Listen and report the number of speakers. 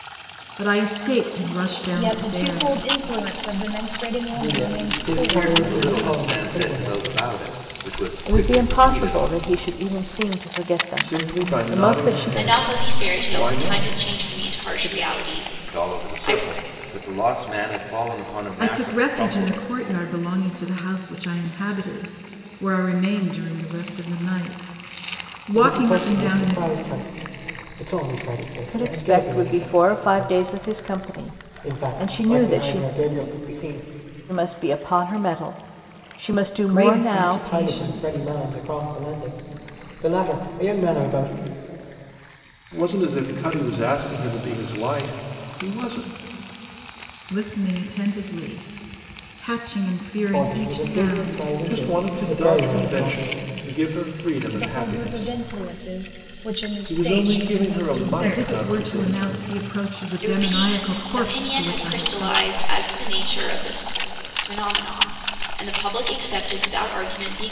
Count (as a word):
seven